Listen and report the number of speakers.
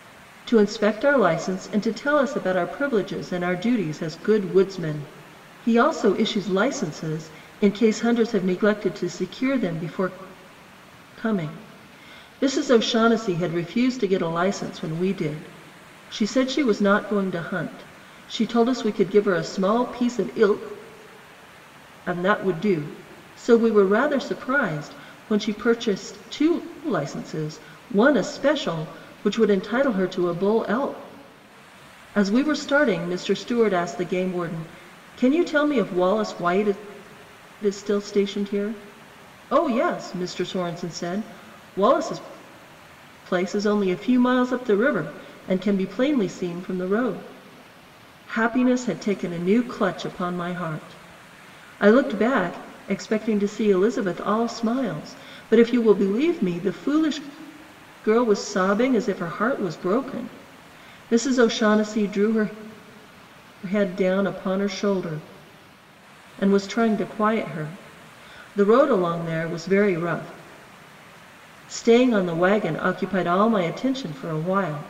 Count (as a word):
one